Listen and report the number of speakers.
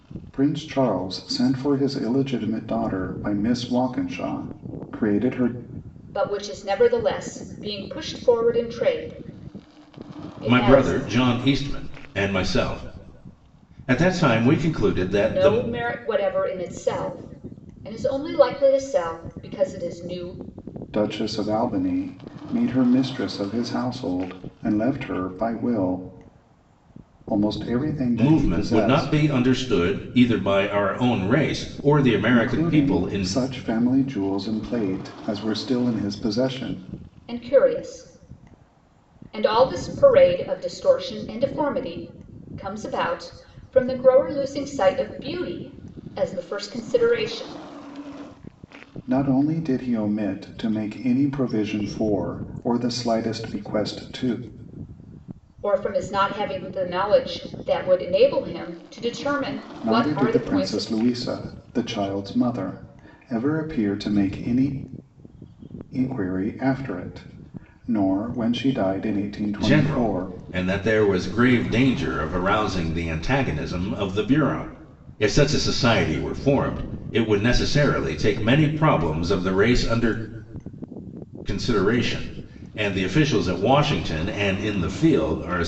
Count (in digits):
3